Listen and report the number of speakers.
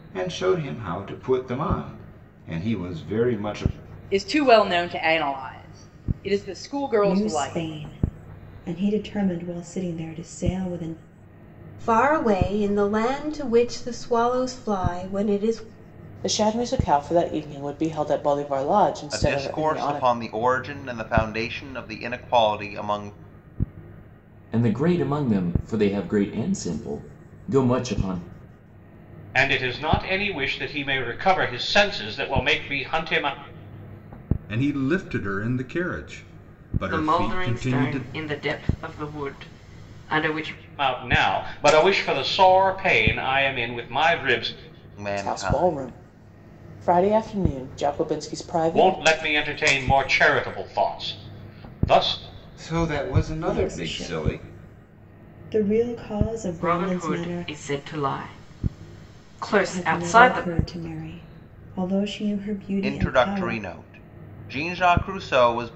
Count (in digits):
10